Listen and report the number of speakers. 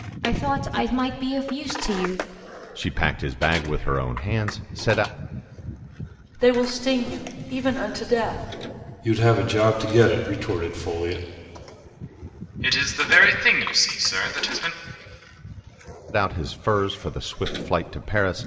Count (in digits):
5